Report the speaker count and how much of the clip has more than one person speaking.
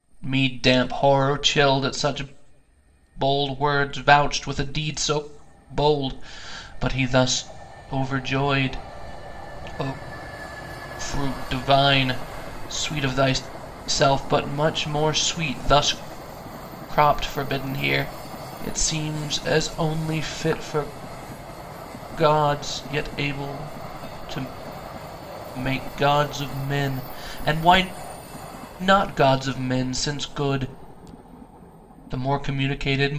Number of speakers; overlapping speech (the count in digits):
1, no overlap